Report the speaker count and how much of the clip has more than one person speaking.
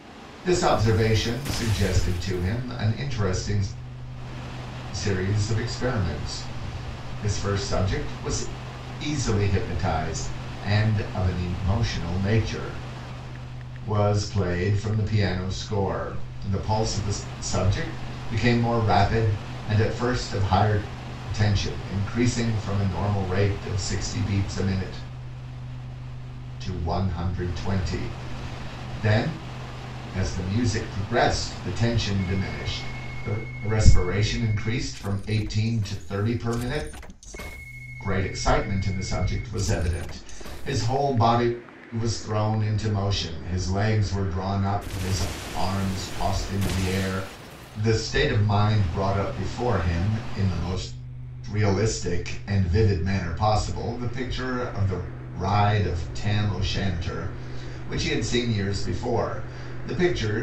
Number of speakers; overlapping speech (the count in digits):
1, no overlap